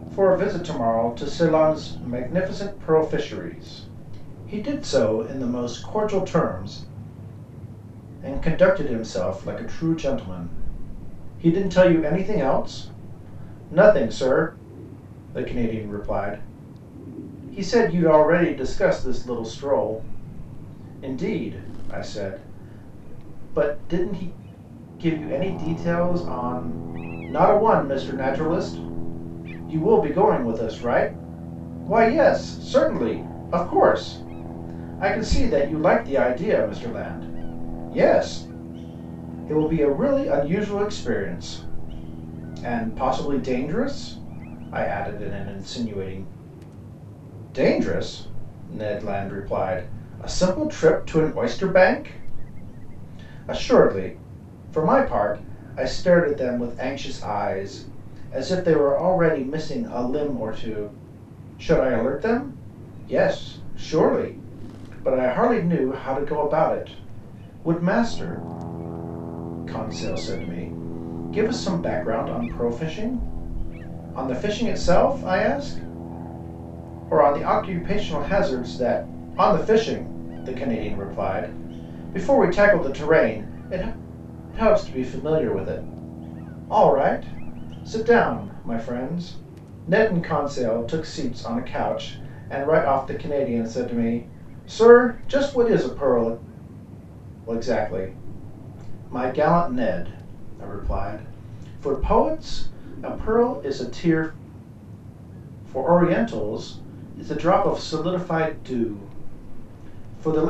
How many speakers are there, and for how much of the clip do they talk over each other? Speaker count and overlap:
1, no overlap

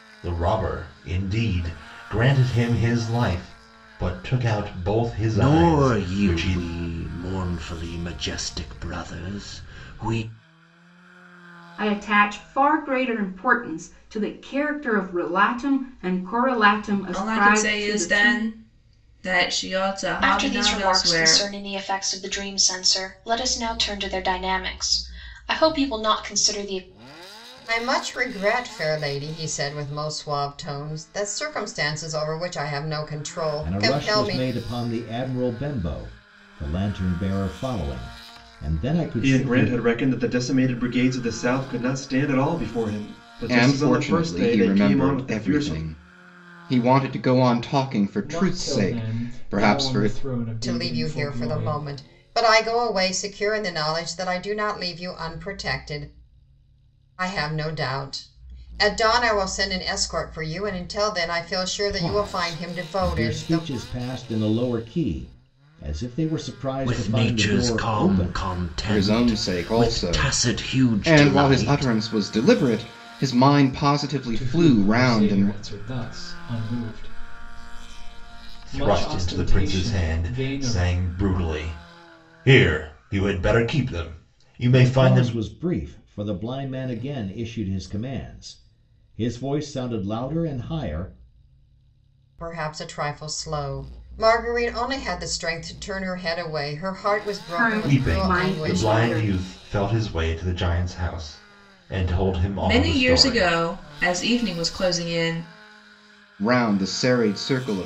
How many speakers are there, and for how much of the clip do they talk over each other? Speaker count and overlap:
10, about 22%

